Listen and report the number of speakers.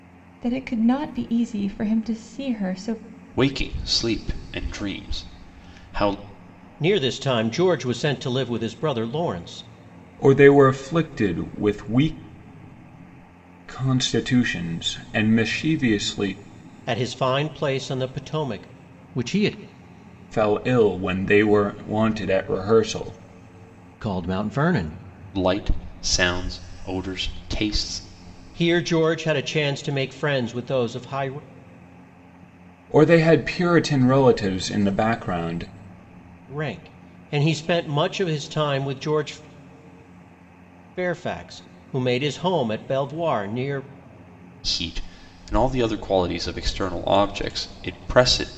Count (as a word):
four